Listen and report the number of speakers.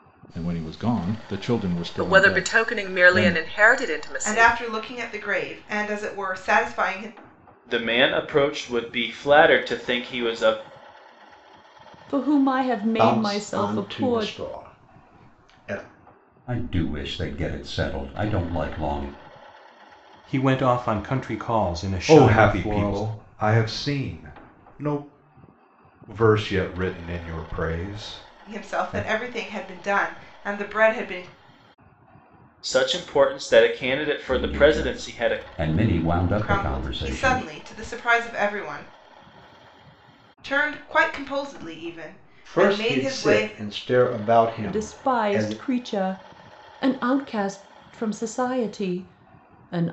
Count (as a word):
nine